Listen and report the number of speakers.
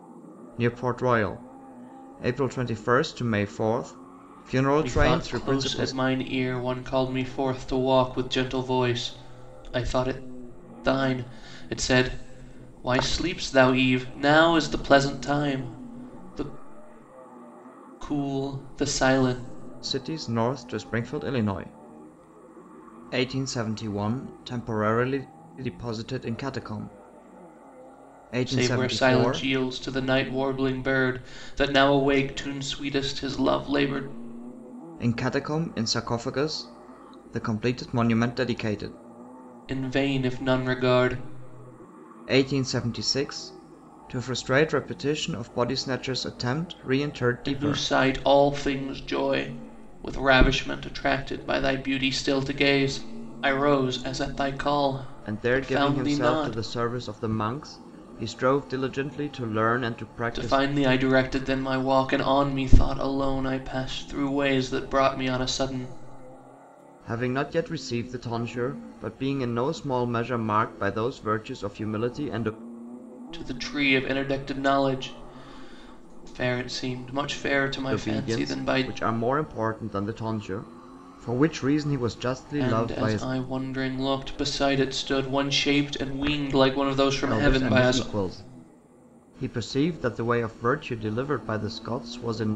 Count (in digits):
2